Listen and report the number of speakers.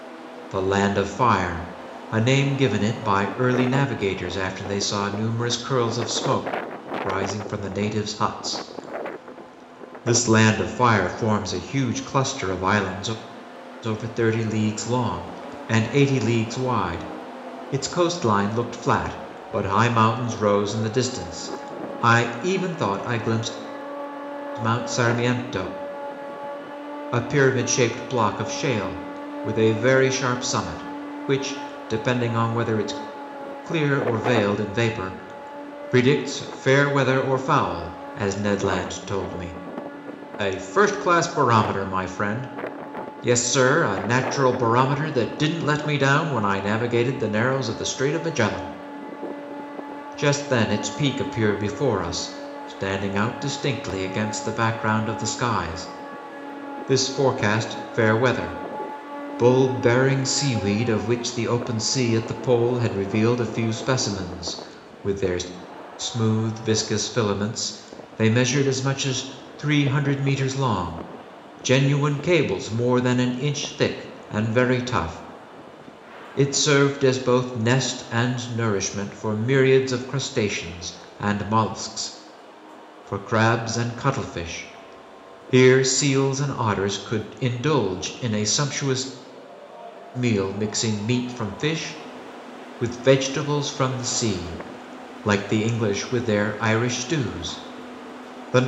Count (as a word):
one